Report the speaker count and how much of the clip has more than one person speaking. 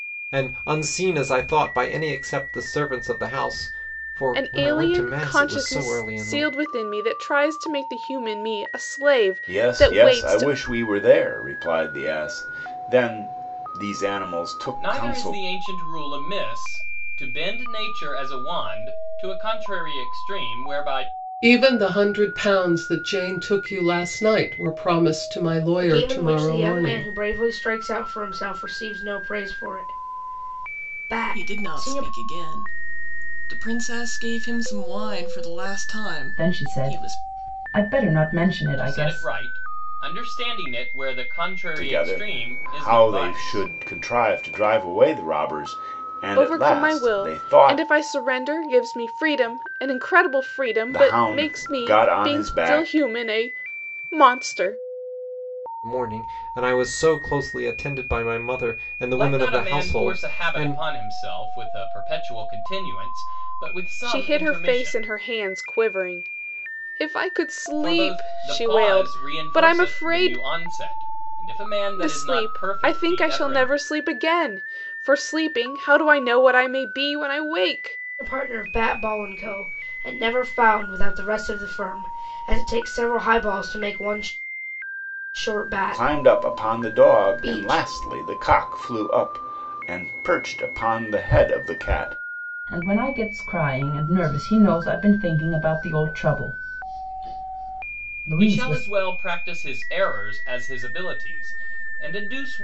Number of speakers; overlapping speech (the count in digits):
8, about 22%